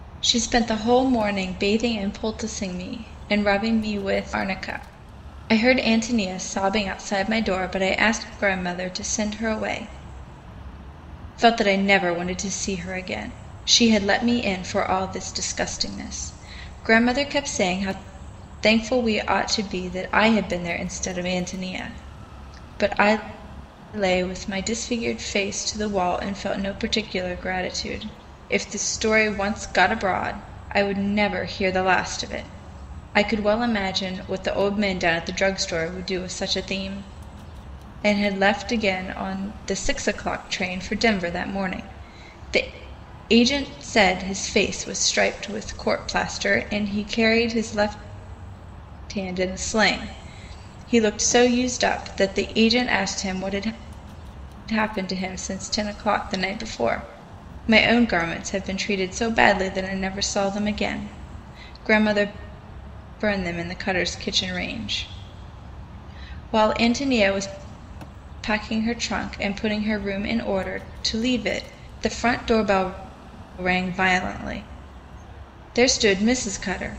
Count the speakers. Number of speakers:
1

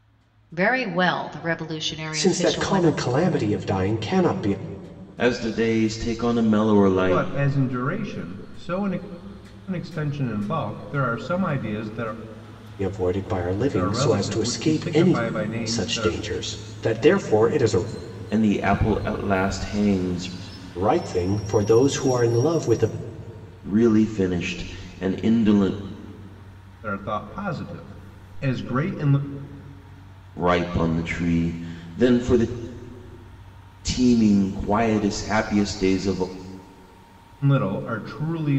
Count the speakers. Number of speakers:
4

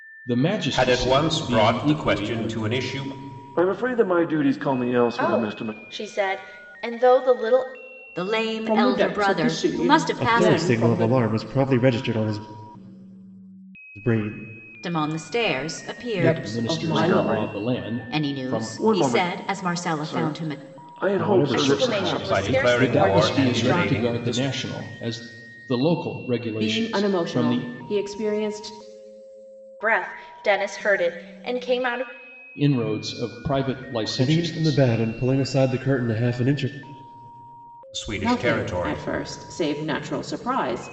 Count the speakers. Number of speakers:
7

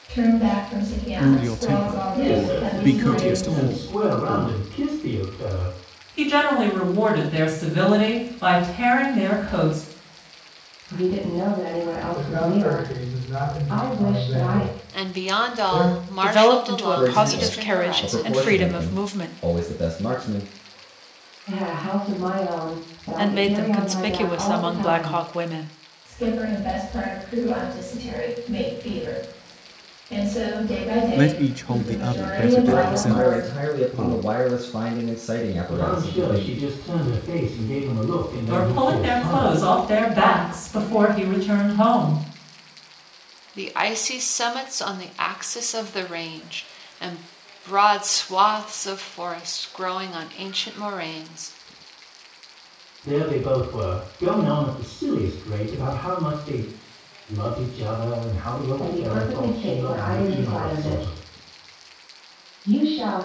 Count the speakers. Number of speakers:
9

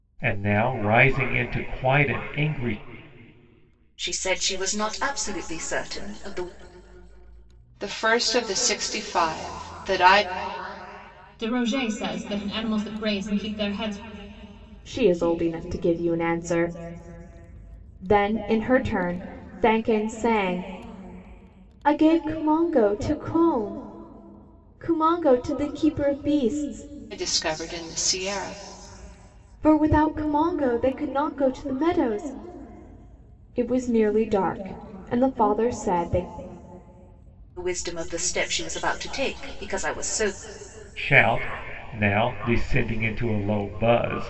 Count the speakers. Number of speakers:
5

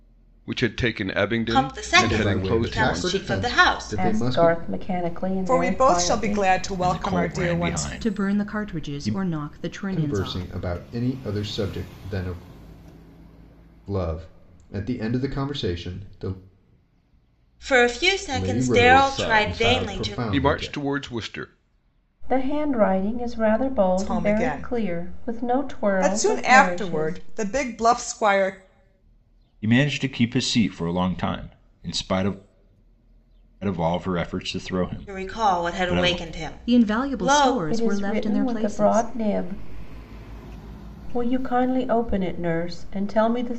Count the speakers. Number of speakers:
7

